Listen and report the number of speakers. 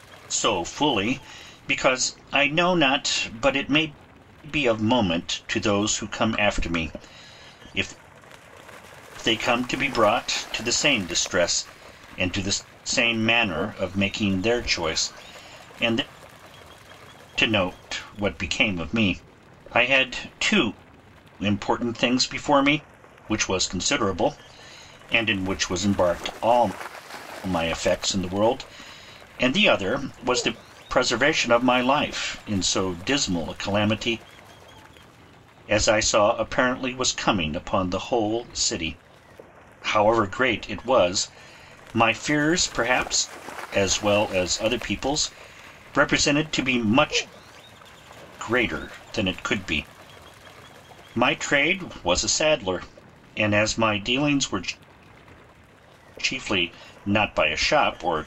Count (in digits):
1